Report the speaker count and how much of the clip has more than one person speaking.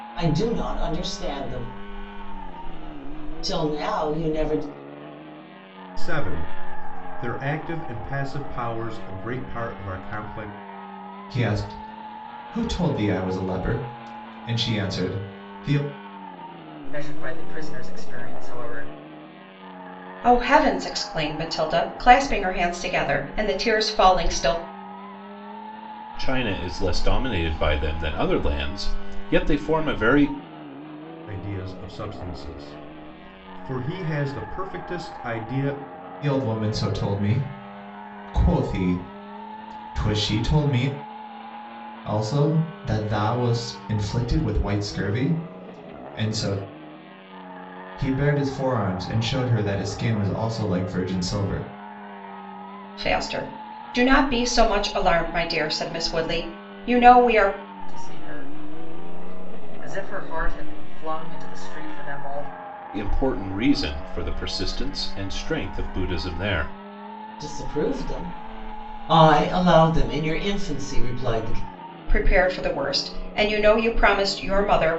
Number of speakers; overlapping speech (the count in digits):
6, no overlap